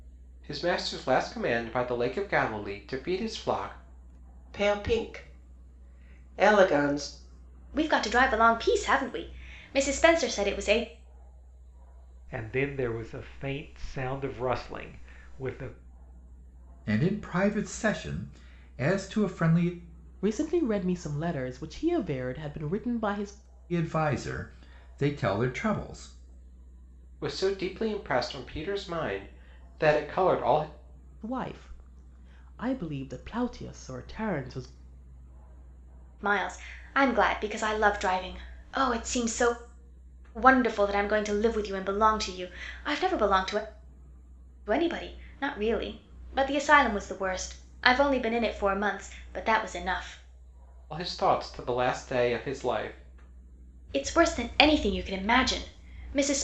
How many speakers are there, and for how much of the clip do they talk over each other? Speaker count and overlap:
6, no overlap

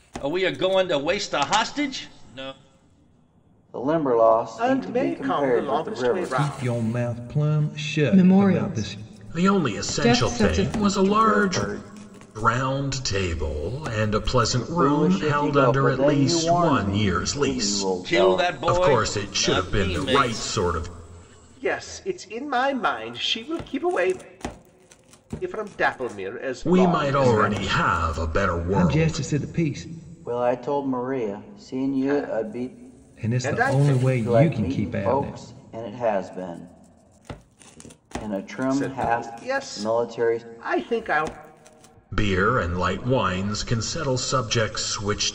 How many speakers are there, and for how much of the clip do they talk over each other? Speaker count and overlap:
6, about 42%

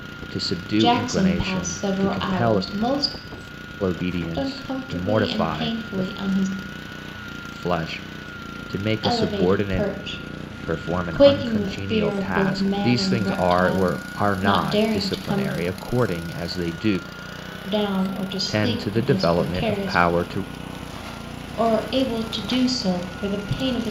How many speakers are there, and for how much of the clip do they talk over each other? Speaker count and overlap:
2, about 45%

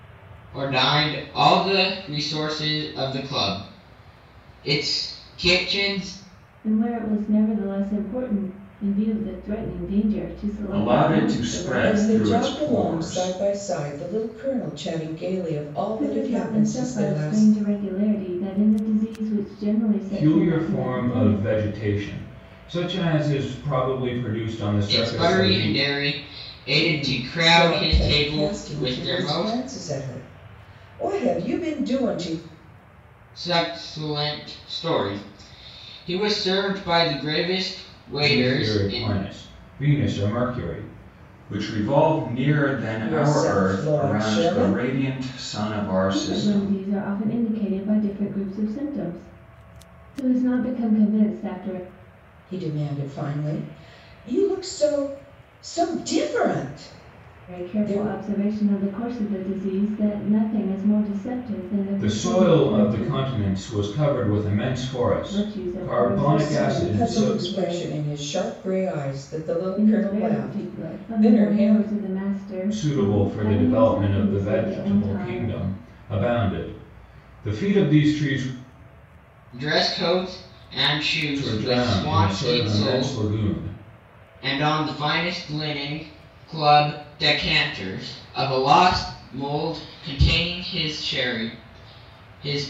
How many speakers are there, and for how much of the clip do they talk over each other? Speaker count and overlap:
4, about 26%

